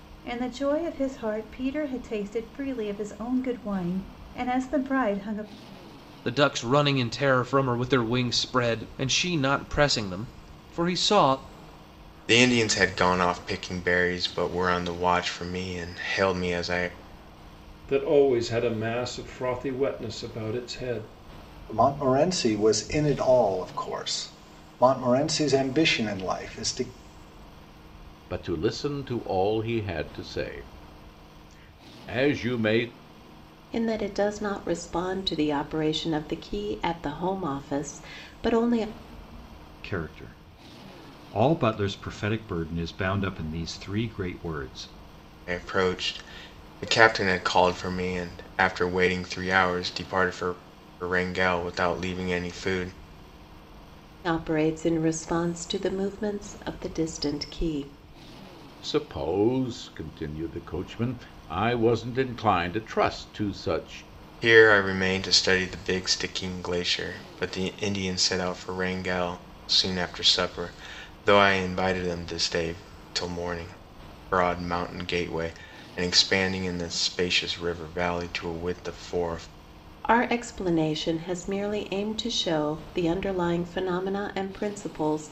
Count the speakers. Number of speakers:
8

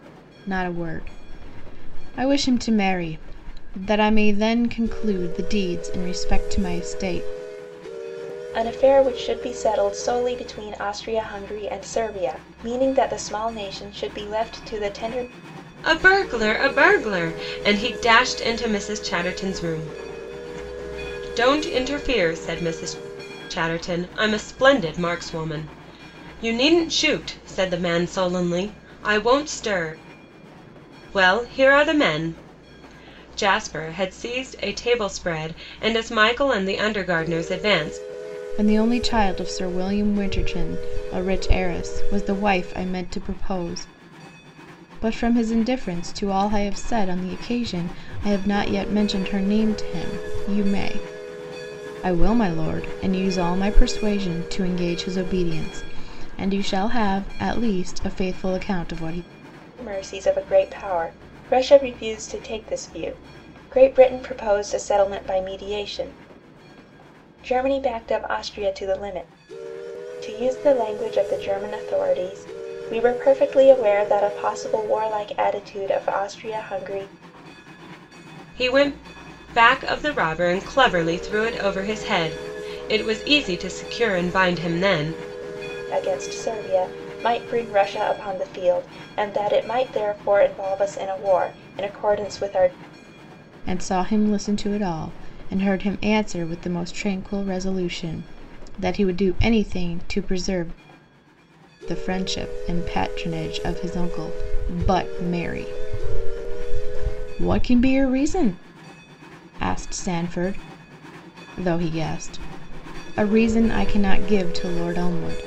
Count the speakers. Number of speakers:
3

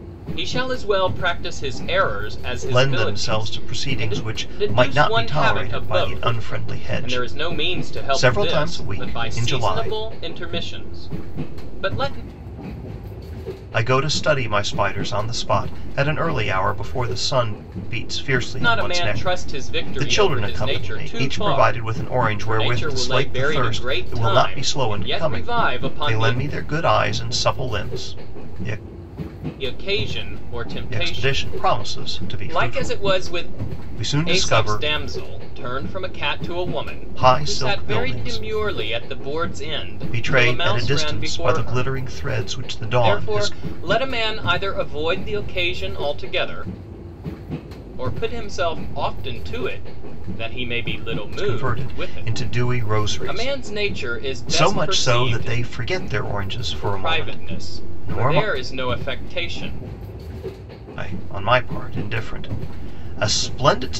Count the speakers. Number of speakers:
2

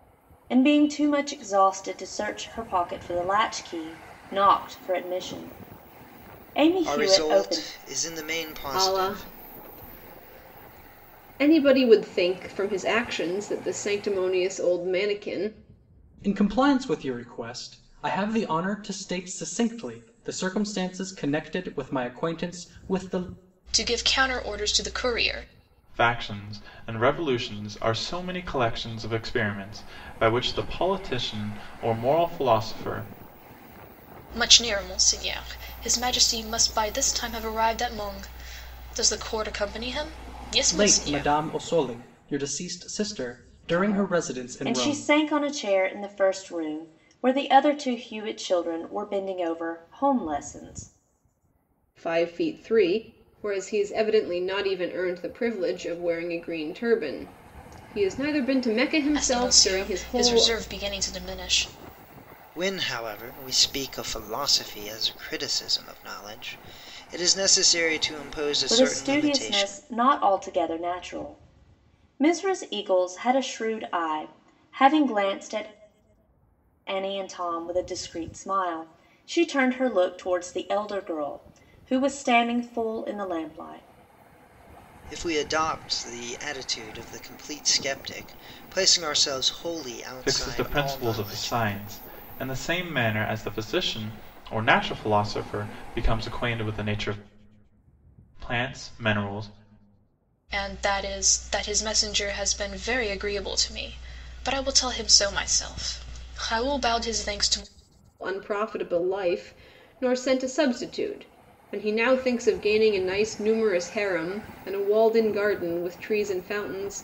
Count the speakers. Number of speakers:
6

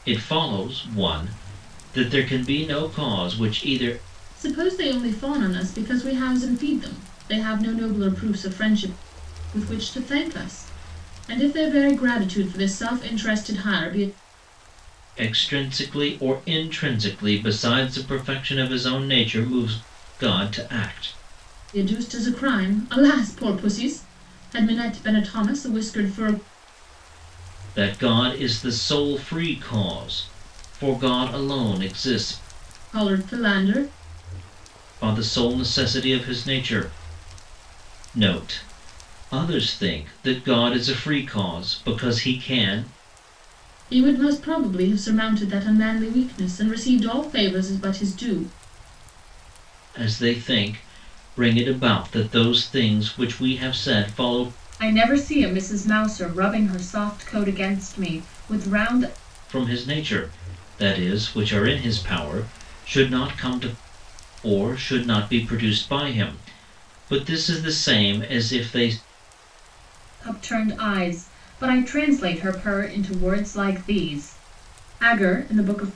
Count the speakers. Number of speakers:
2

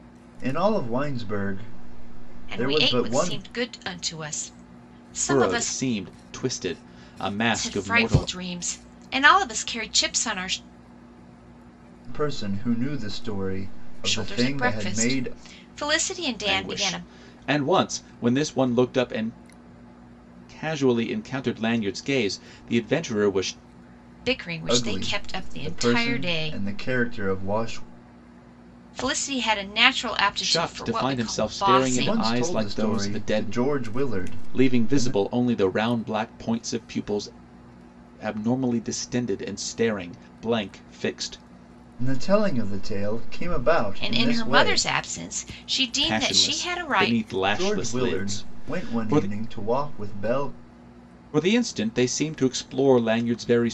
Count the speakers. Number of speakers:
3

